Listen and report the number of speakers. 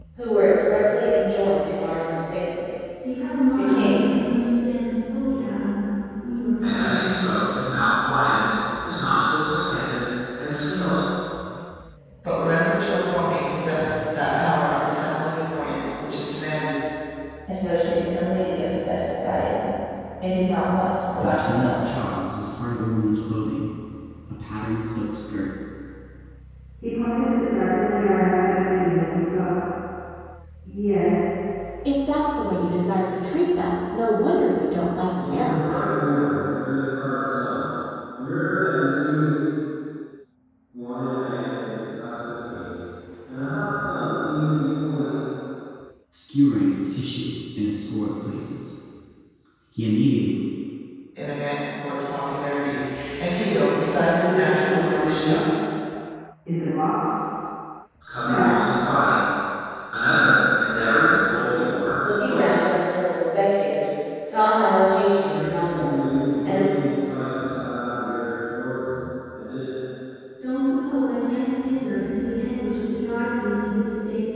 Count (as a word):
nine